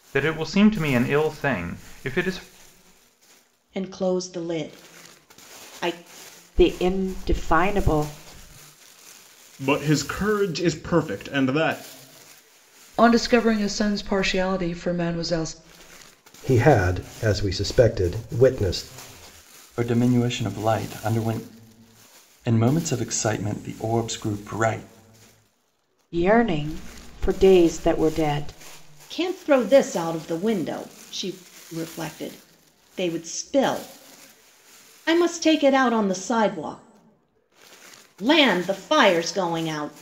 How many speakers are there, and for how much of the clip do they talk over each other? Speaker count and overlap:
7, no overlap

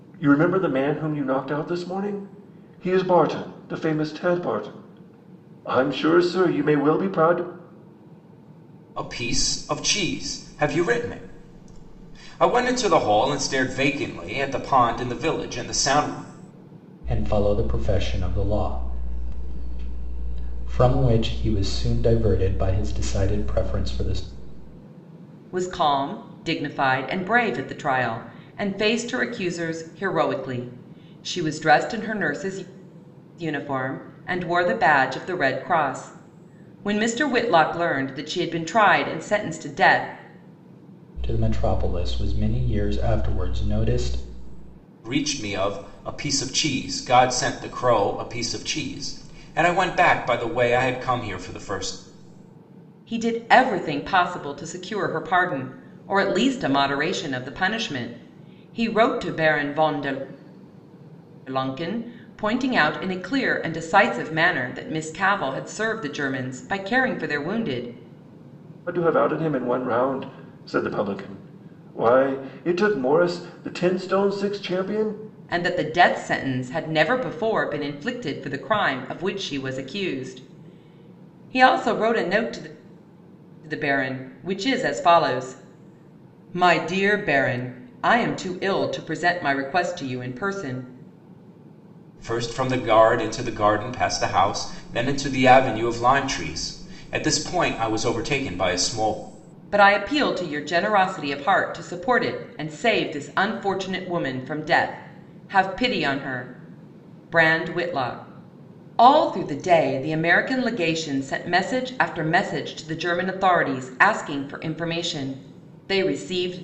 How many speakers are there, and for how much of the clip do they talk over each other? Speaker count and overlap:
4, no overlap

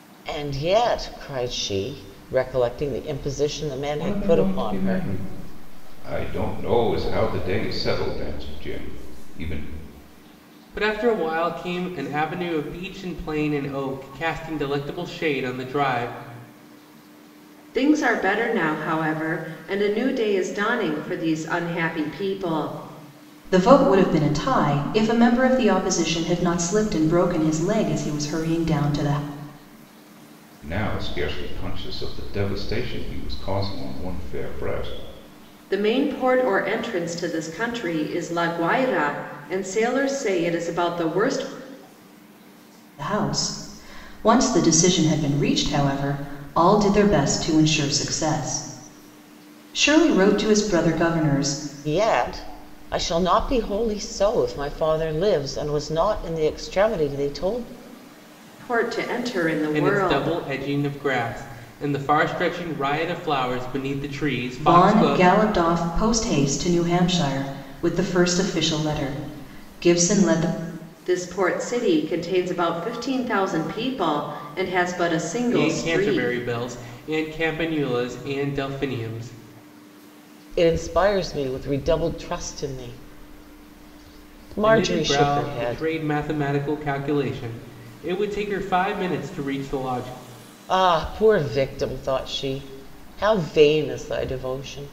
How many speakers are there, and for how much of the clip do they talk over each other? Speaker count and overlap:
5, about 5%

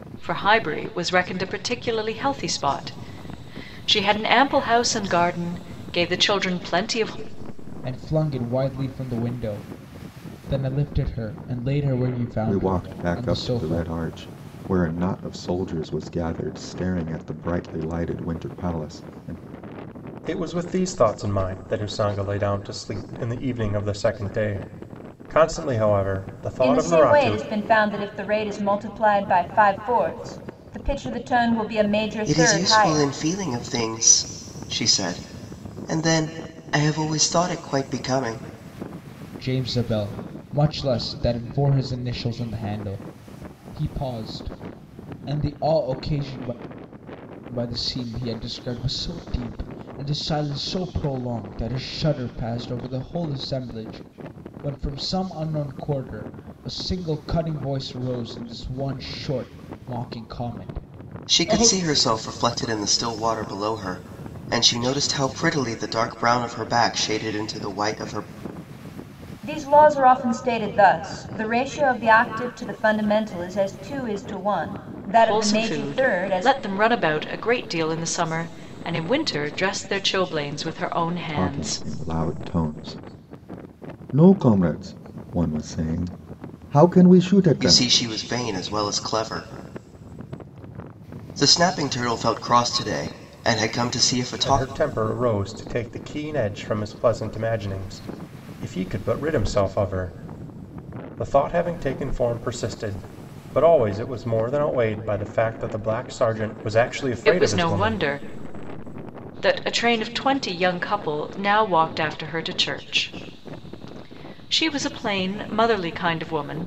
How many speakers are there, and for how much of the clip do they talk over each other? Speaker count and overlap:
6, about 6%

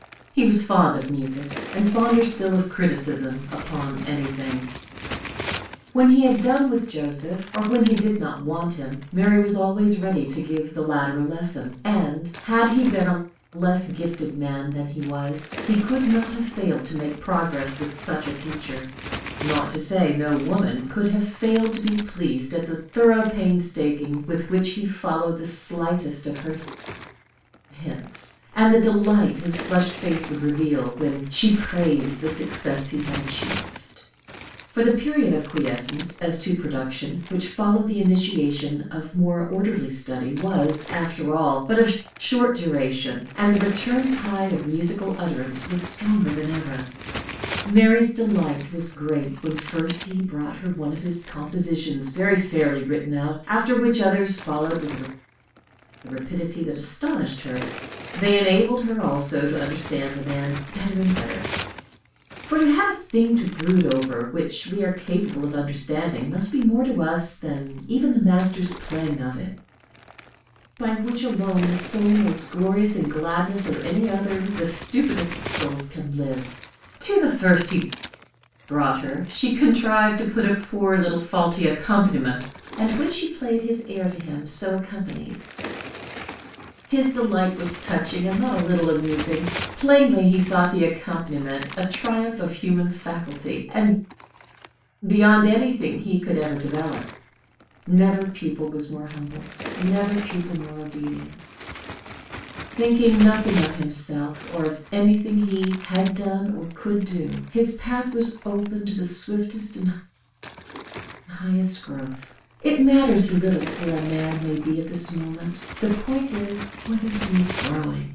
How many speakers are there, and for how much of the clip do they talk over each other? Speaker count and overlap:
1, no overlap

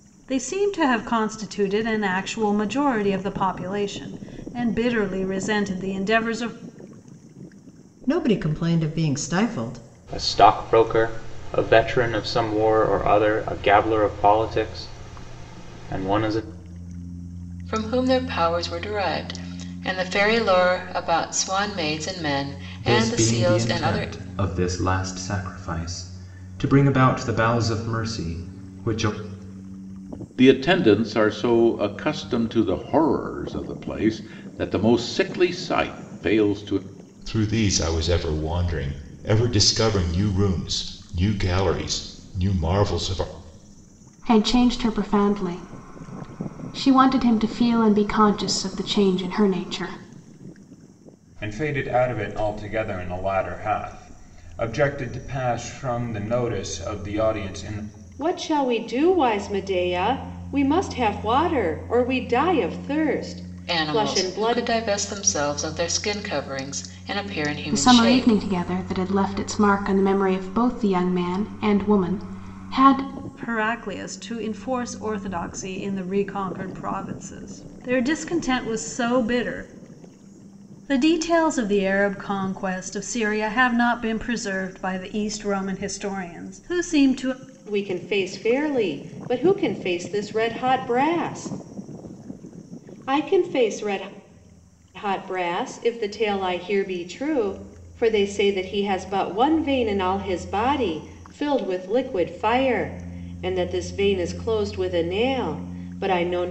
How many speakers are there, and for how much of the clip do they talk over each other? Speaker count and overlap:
10, about 3%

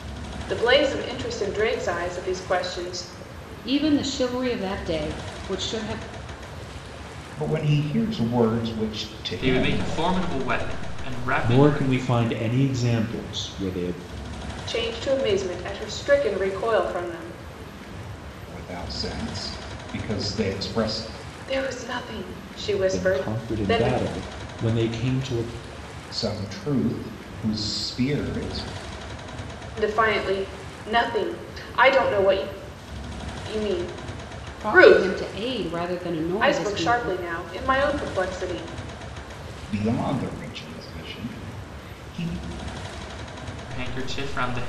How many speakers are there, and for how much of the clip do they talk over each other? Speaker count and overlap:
5, about 8%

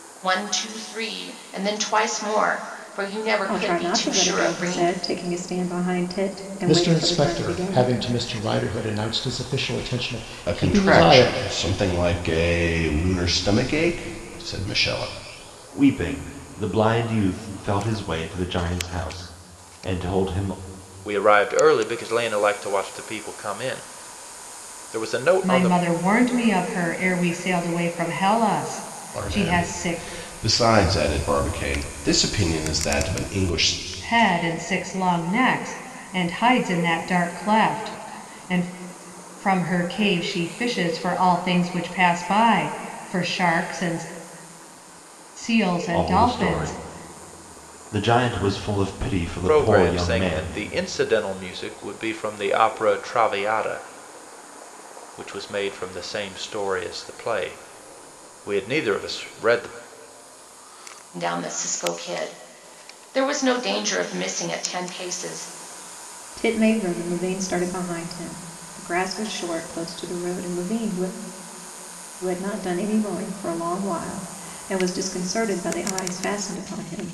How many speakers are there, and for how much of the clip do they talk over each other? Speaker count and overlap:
7, about 9%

